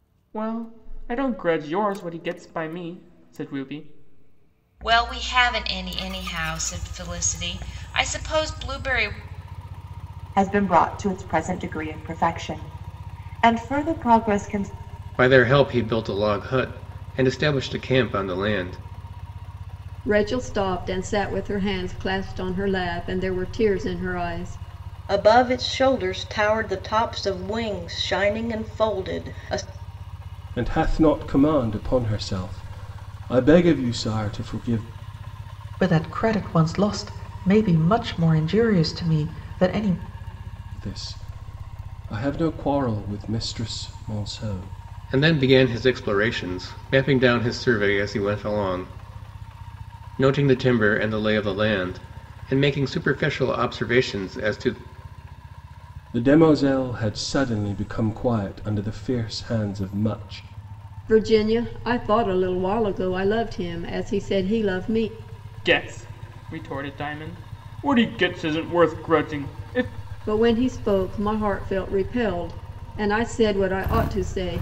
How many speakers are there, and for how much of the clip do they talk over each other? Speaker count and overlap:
eight, no overlap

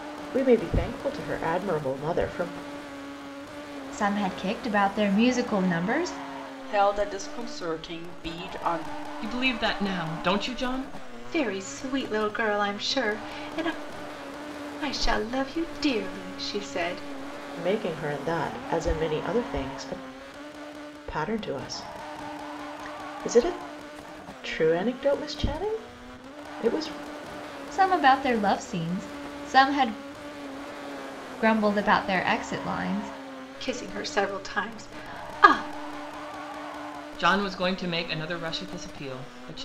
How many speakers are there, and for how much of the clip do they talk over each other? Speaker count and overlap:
five, no overlap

